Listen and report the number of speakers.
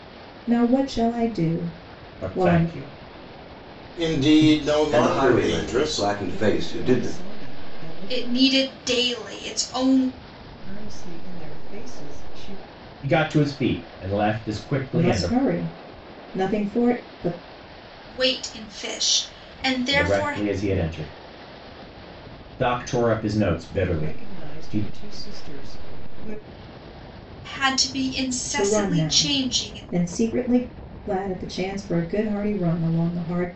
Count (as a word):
six